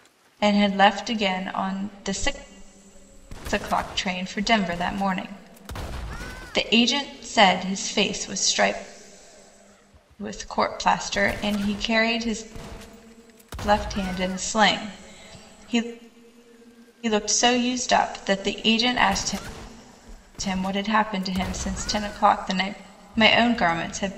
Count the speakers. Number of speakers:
one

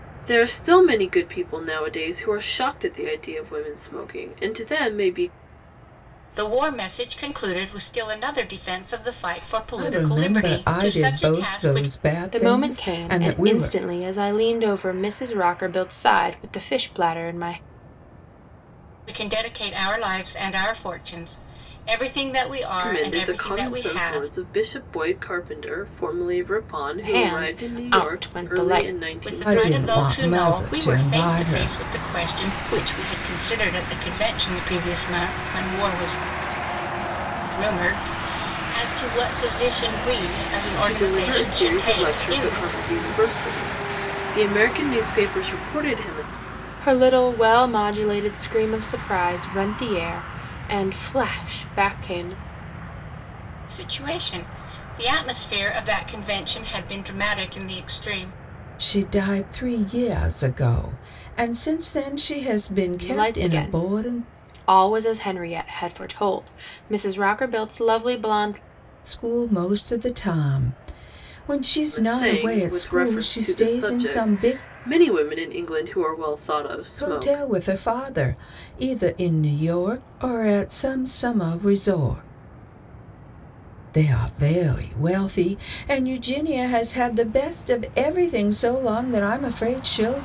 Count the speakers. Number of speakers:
four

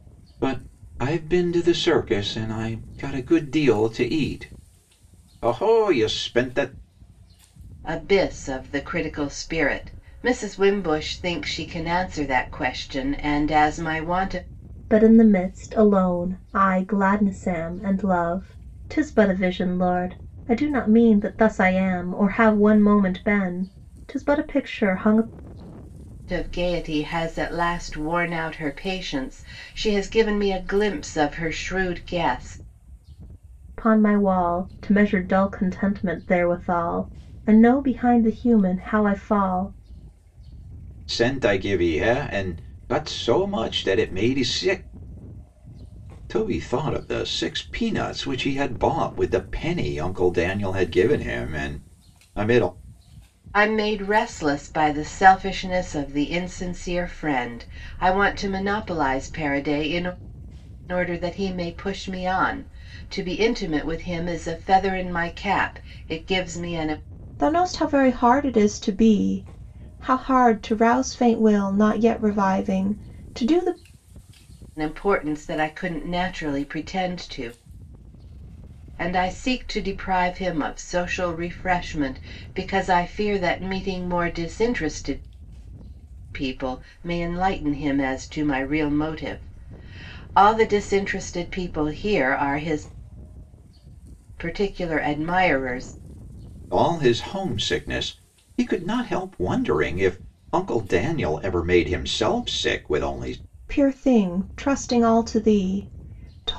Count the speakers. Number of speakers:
three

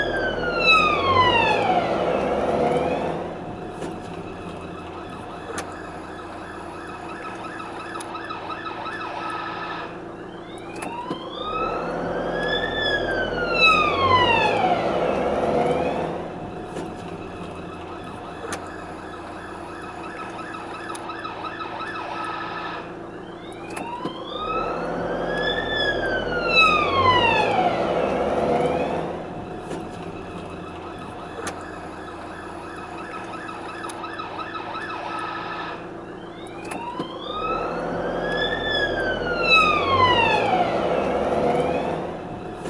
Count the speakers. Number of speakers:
zero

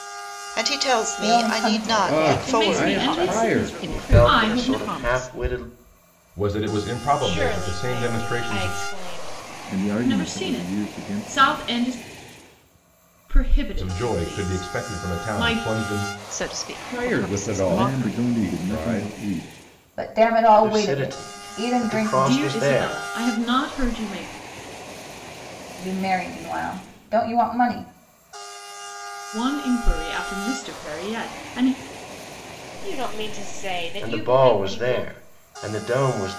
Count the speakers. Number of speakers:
nine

